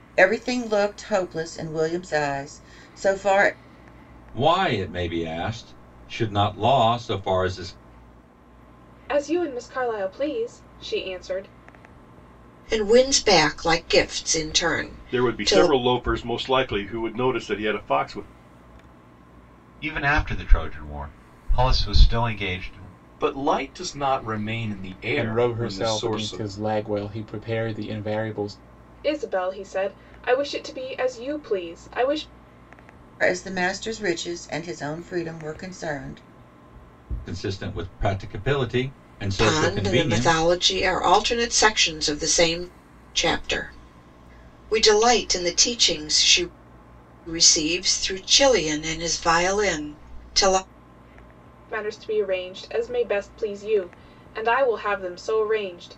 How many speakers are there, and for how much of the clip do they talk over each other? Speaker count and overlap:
8, about 6%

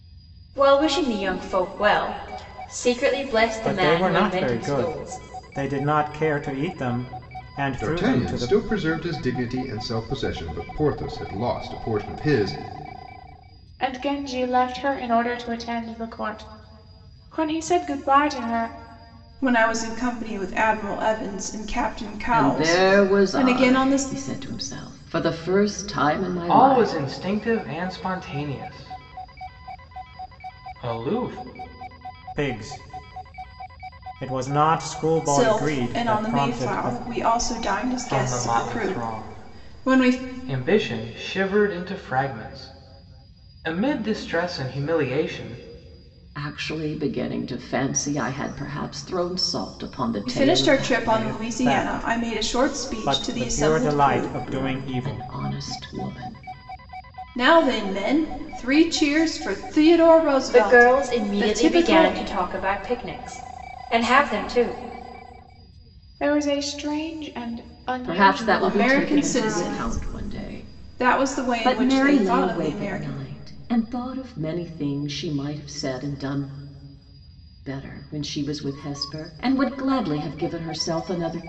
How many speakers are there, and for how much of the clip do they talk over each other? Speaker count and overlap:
7, about 24%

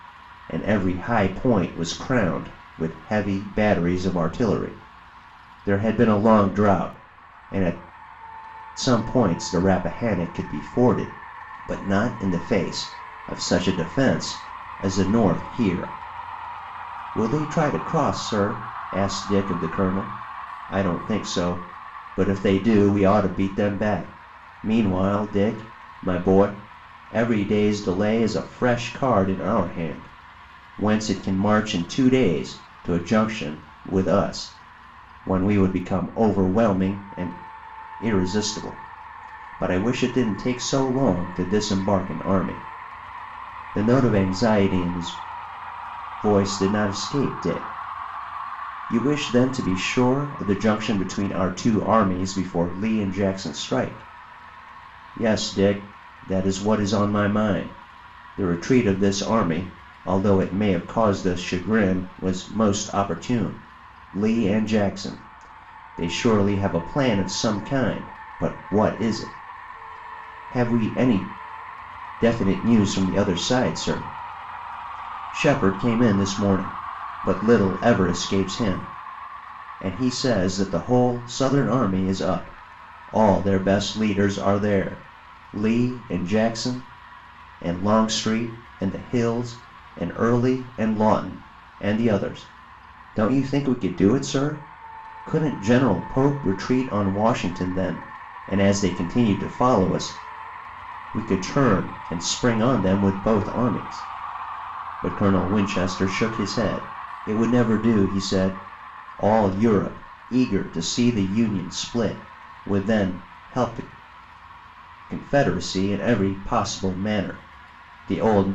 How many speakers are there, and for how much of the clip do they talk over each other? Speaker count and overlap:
1, no overlap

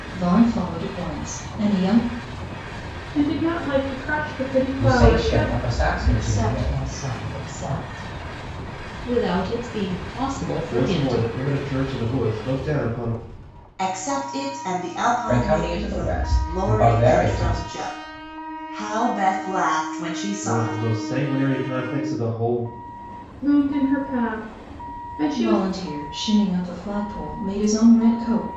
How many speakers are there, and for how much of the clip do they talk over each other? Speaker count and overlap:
7, about 18%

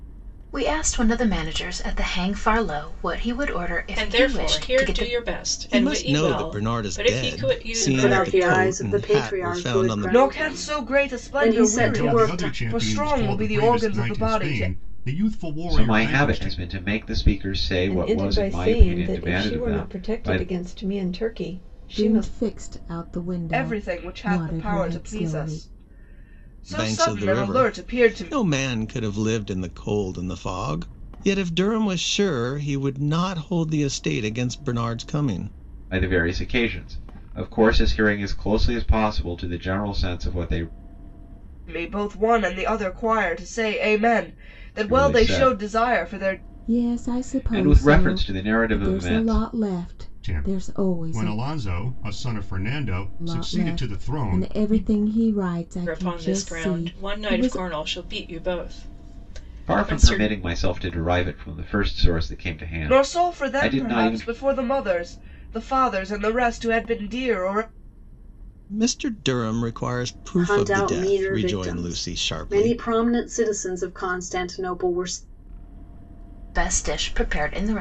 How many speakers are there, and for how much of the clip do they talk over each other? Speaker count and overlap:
9, about 41%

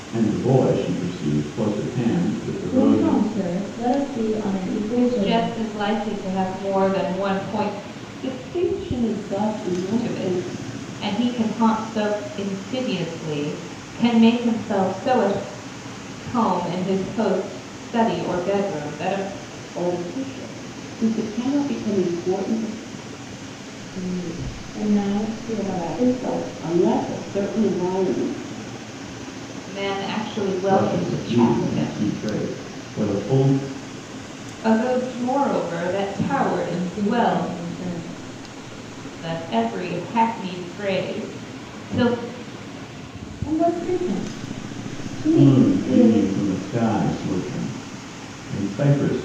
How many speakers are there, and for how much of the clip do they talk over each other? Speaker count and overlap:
4, about 14%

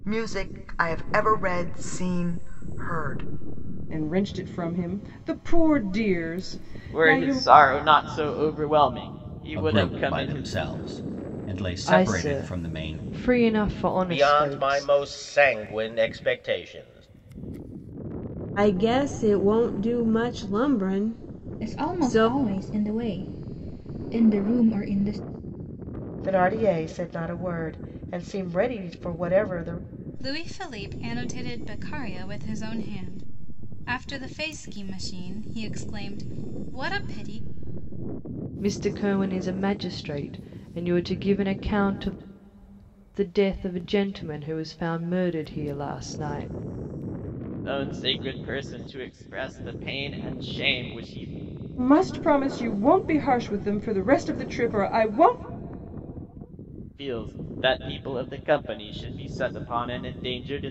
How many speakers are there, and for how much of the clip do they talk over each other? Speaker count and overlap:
10, about 7%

